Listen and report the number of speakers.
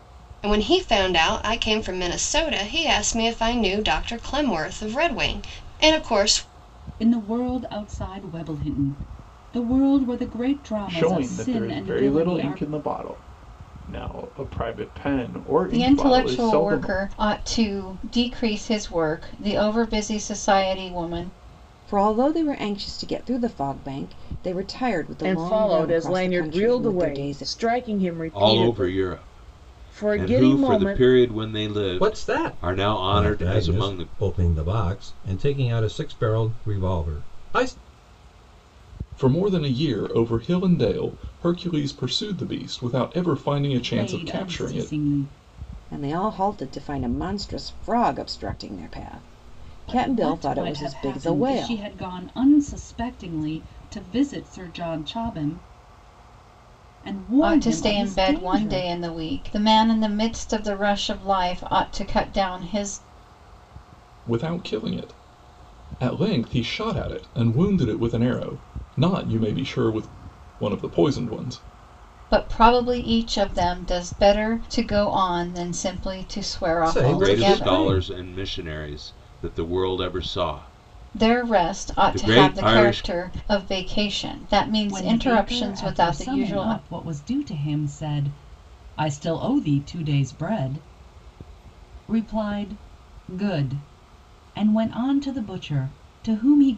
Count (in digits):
9